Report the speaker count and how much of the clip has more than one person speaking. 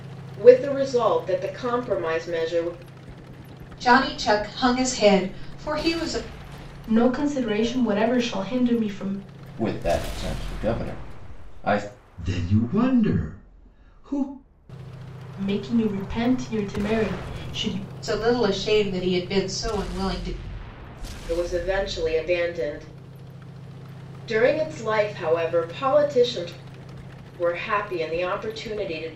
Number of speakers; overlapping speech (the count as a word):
five, no overlap